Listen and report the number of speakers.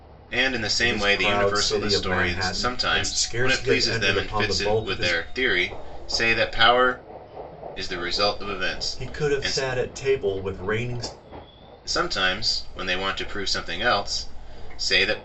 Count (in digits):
2